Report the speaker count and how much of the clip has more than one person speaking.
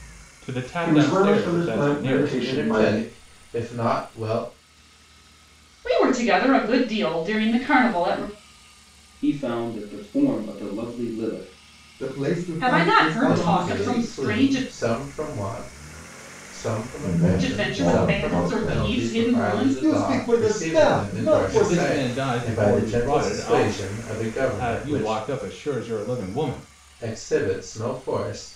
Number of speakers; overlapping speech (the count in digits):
6, about 41%